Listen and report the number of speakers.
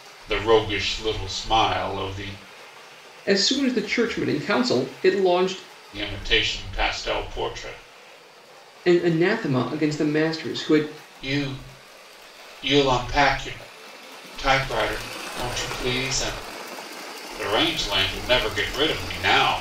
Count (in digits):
2